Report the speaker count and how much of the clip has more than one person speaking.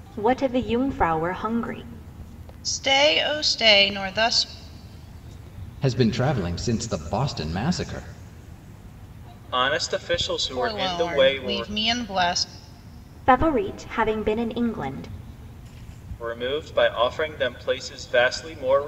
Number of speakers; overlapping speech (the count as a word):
four, about 7%